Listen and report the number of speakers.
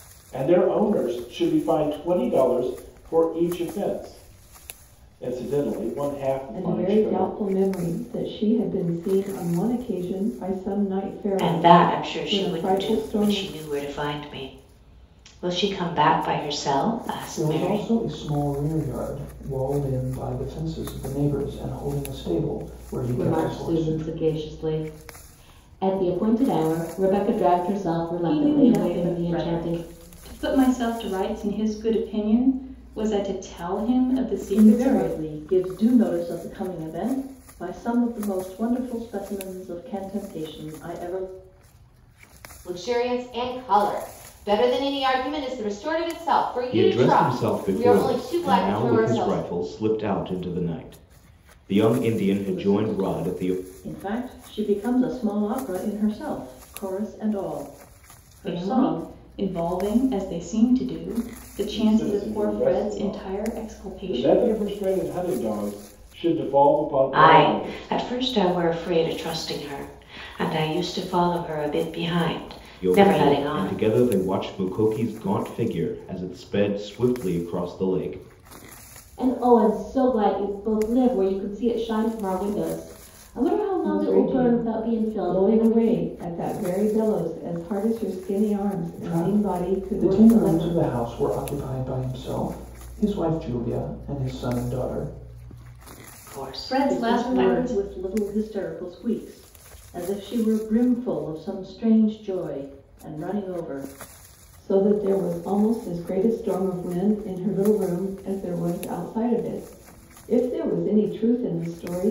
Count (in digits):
9